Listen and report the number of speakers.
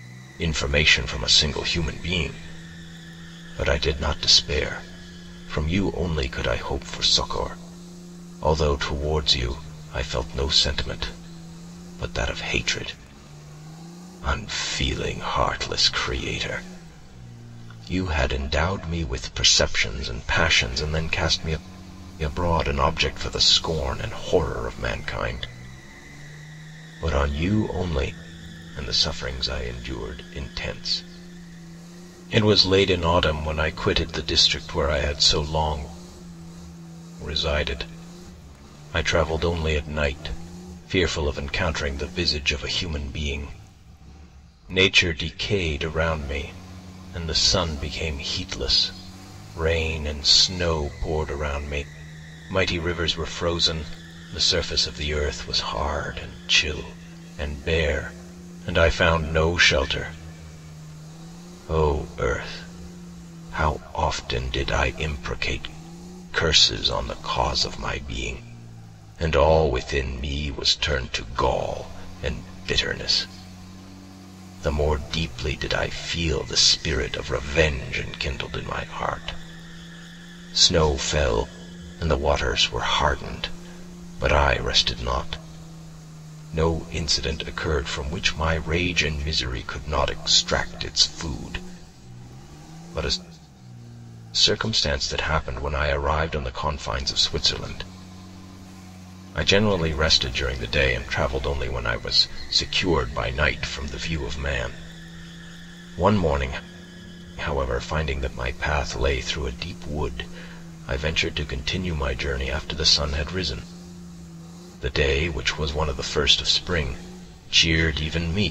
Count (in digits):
1